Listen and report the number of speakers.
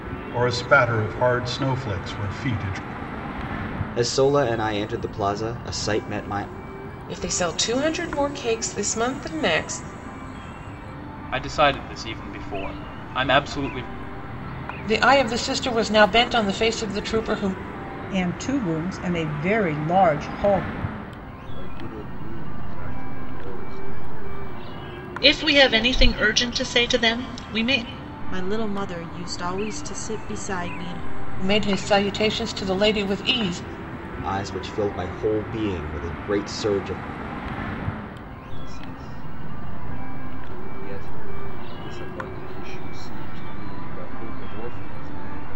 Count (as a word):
nine